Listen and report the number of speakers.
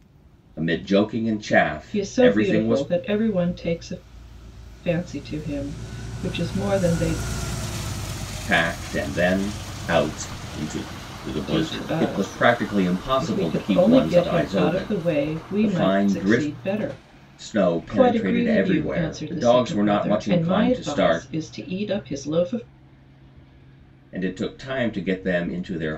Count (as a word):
two